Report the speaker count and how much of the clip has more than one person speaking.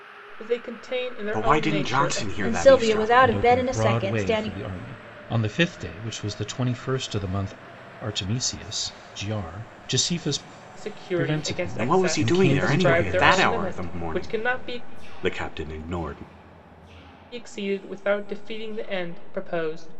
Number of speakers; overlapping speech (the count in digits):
4, about 35%